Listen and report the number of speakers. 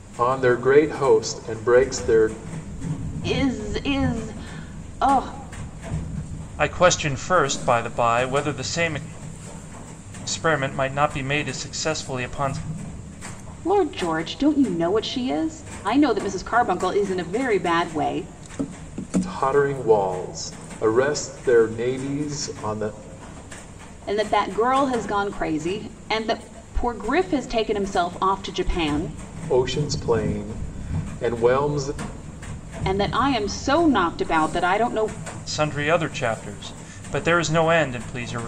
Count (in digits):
3